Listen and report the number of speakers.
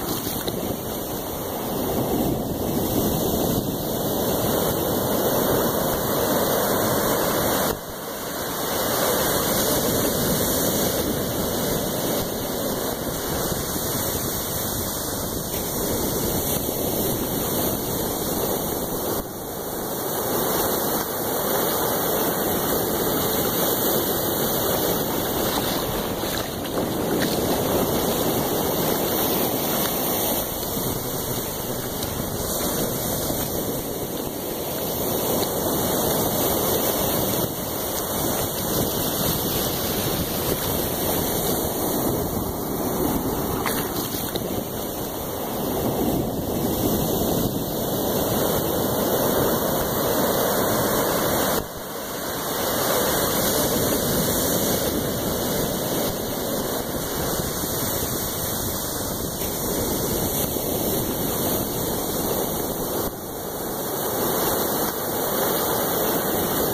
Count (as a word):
zero